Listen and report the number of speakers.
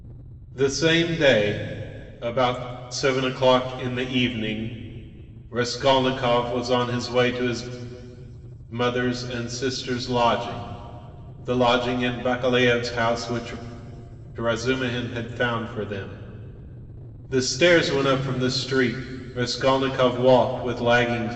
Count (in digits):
1